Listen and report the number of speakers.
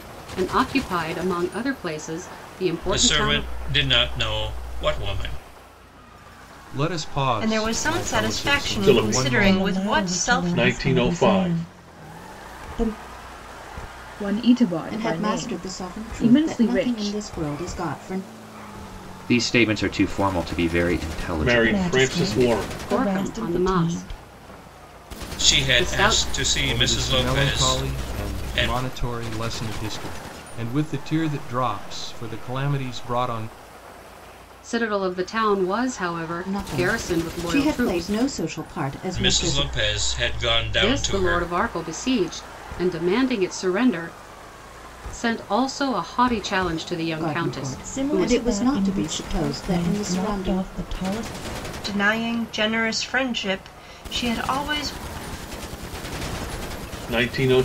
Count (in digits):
9